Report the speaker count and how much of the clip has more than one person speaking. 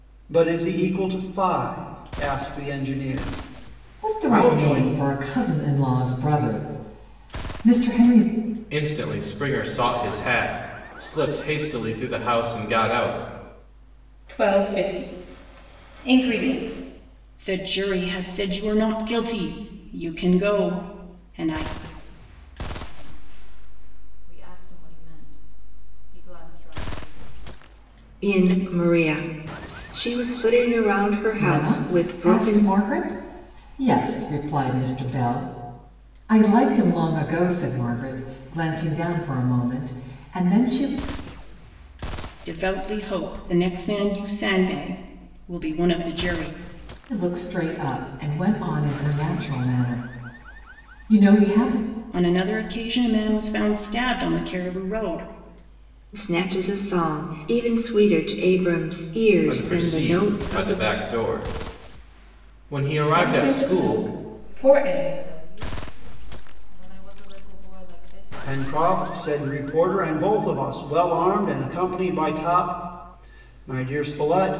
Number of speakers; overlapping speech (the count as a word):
seven, about 8%